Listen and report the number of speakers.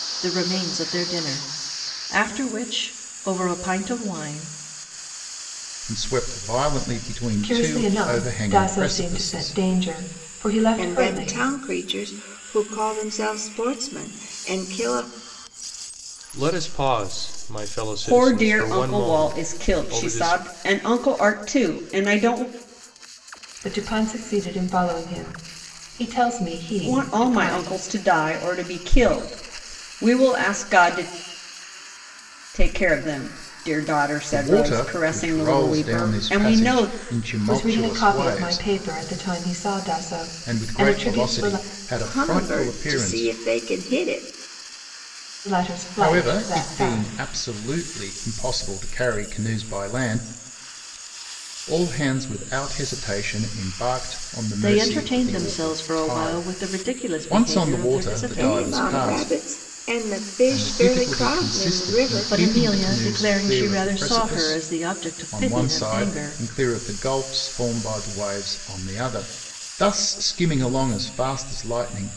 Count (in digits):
6